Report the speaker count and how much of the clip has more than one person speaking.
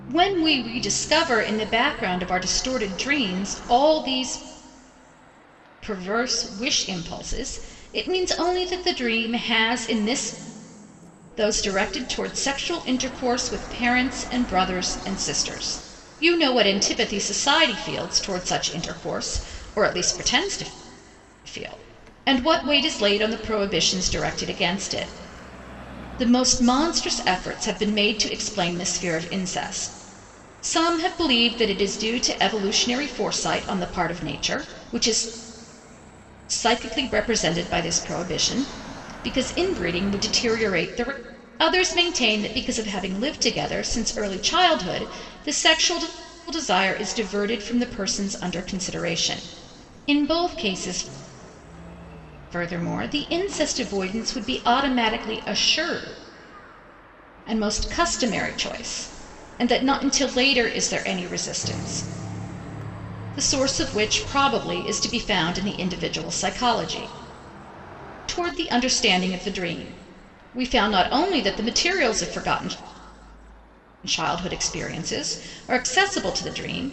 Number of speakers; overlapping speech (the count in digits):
1, no overlap